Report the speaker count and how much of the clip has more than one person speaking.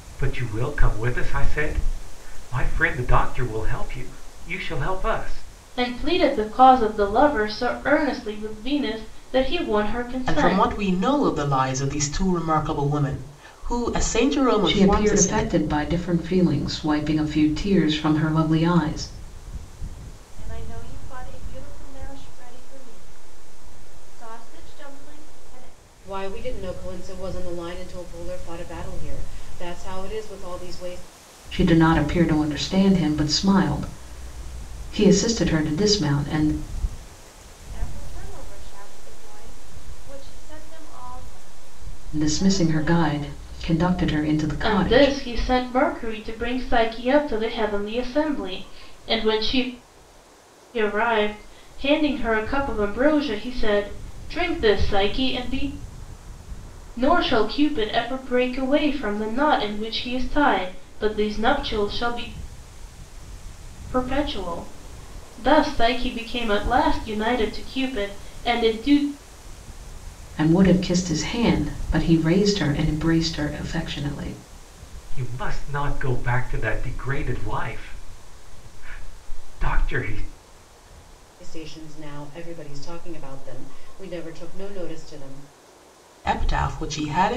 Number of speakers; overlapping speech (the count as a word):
six, about 3%